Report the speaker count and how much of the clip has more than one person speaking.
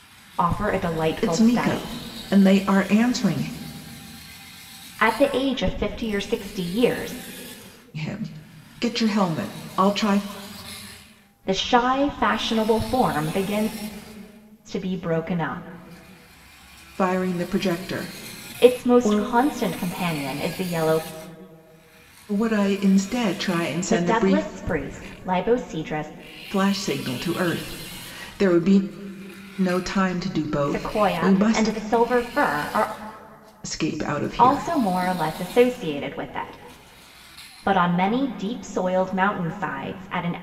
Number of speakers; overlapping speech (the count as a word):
two, about 9%